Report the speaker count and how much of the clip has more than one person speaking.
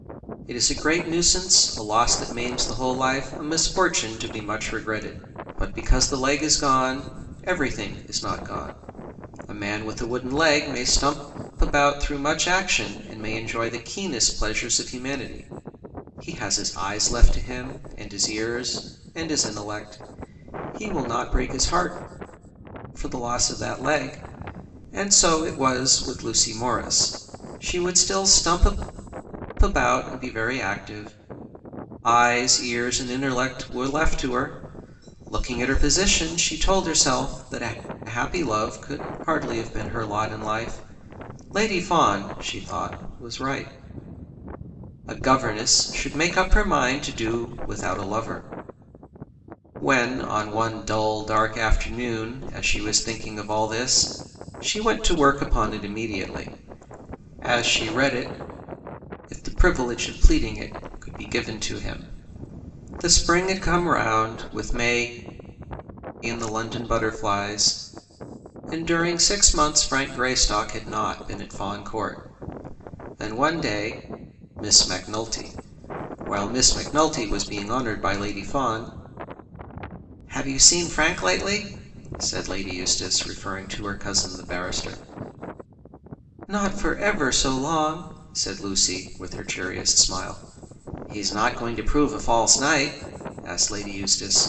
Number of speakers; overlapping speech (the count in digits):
1, no overlap